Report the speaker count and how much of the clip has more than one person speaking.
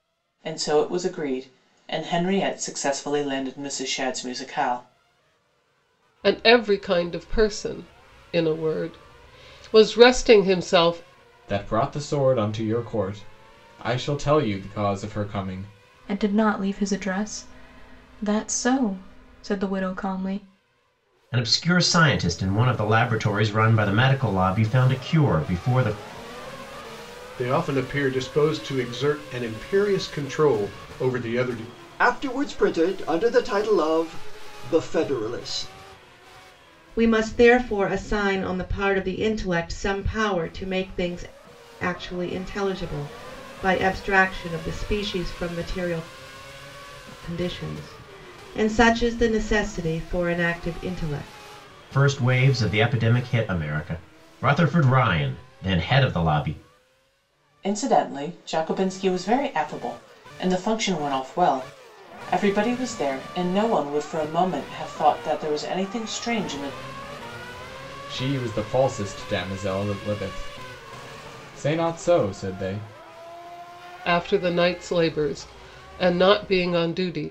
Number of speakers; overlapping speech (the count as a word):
eight, no overlap